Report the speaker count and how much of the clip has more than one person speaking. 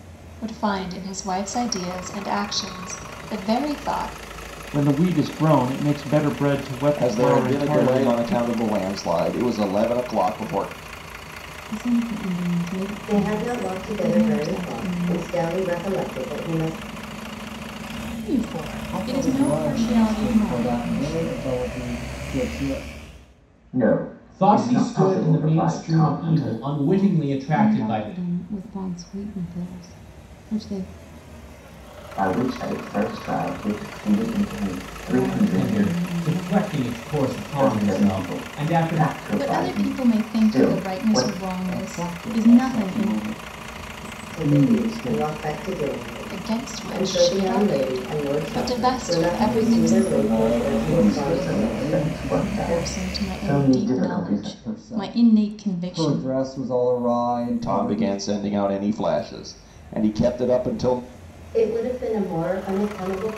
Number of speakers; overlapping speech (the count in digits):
9, about 44%